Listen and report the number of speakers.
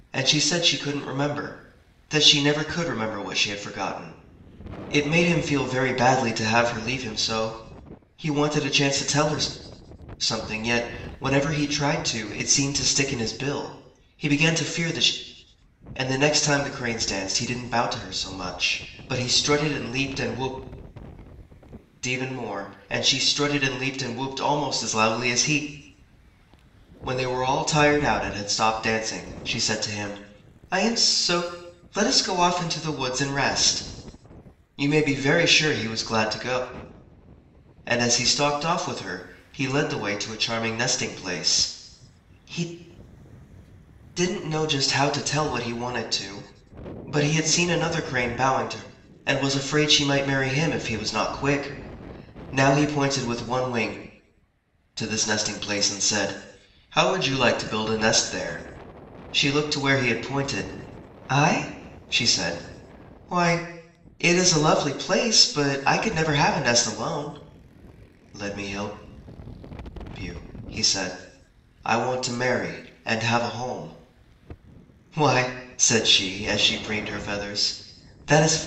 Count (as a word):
one